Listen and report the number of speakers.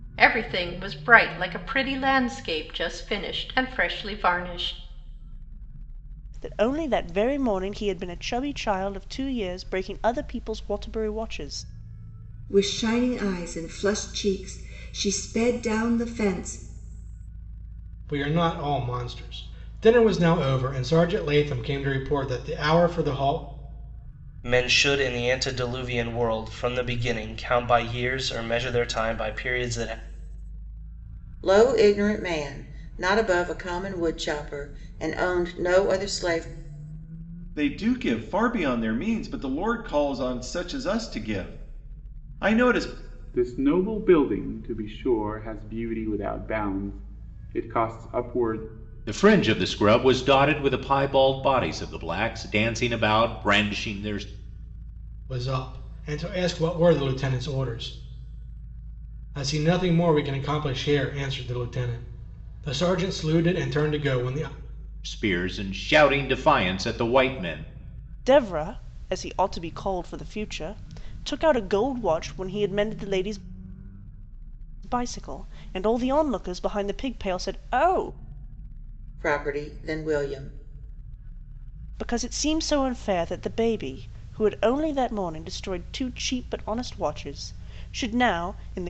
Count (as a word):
nine